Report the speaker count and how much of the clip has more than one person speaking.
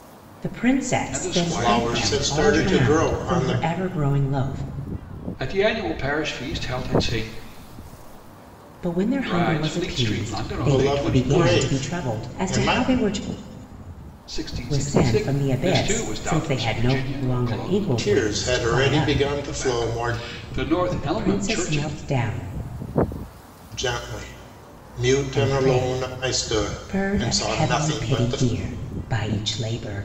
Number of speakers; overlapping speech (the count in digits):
3, about 51%